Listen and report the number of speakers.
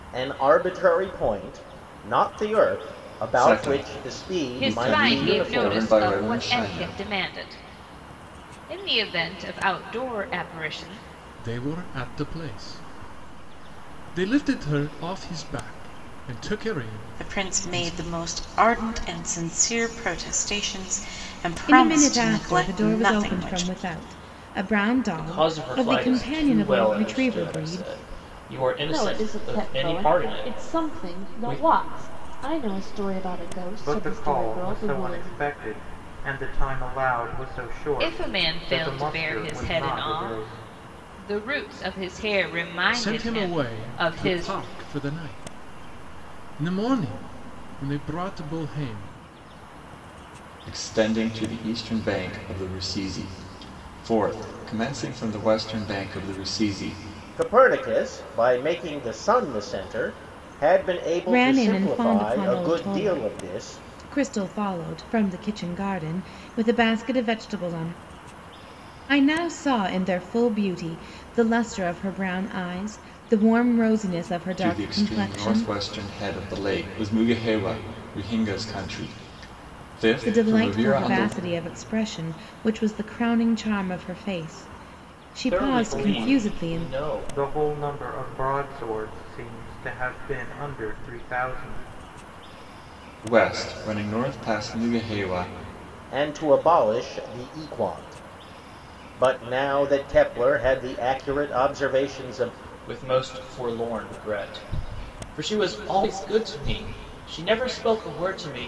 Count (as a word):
nine